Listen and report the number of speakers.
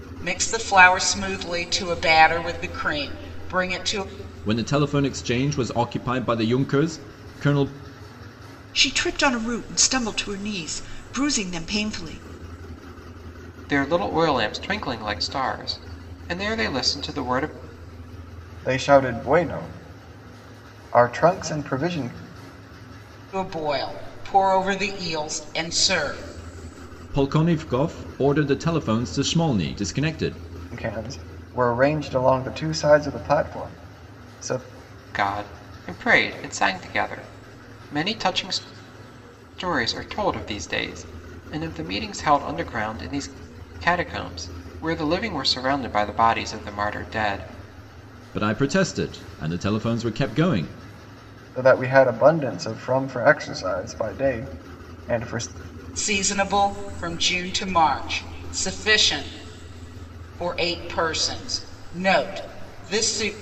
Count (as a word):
five